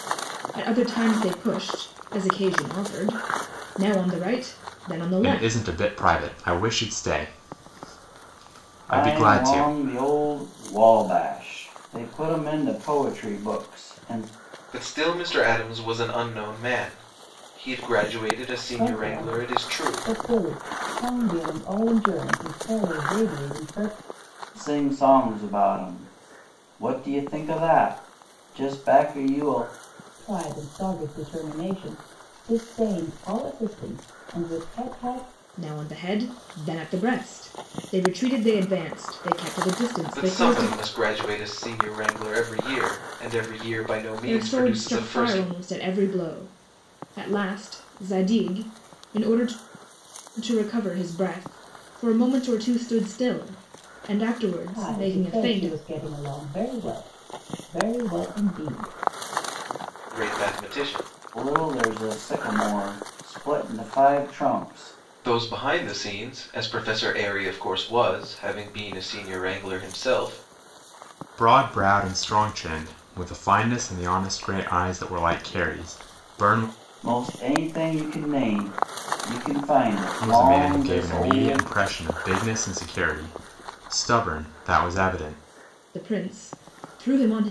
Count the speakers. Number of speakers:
5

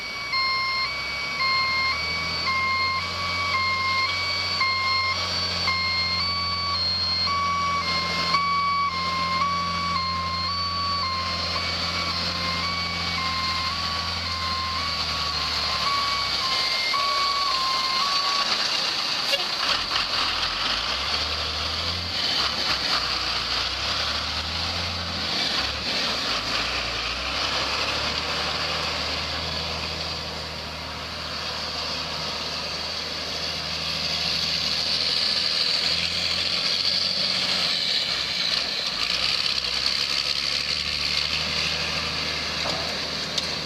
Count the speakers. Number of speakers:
0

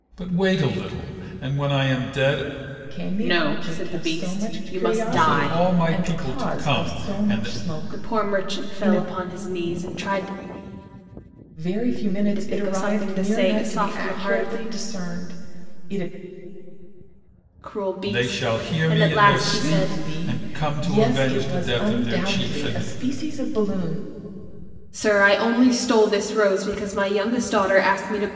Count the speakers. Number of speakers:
3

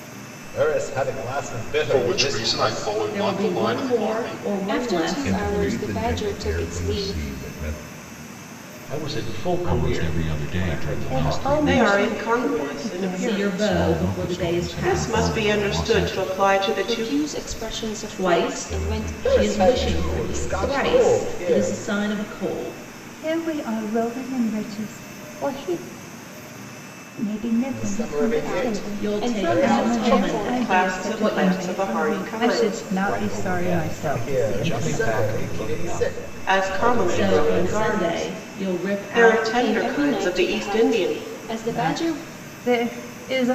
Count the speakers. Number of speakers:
9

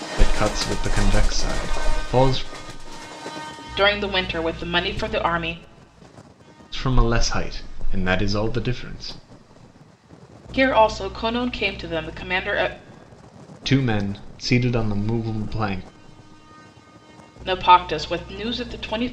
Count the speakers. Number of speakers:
2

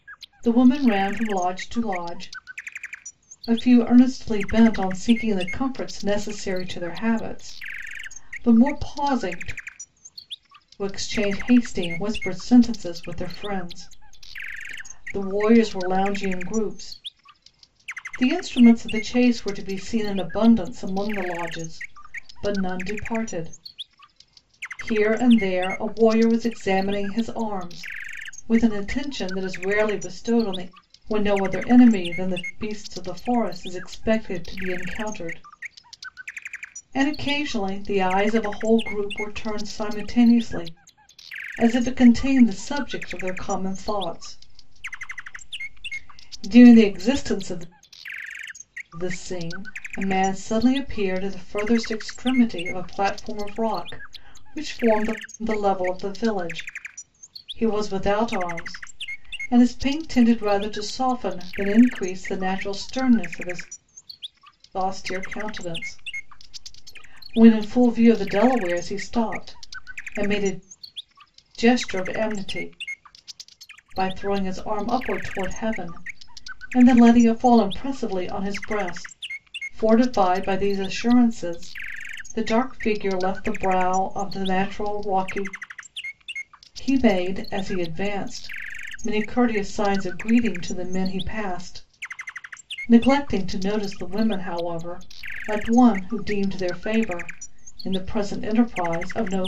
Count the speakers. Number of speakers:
1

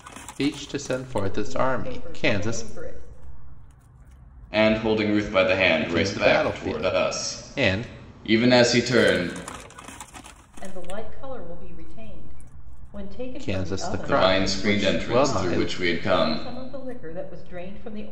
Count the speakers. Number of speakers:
3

